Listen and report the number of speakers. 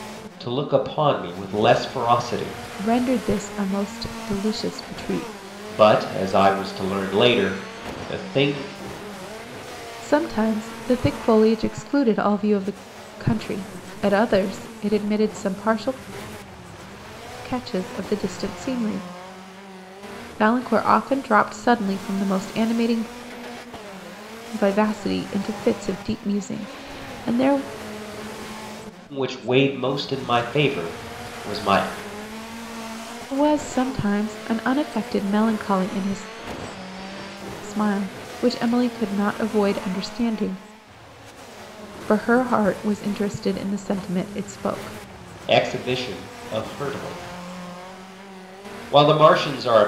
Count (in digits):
2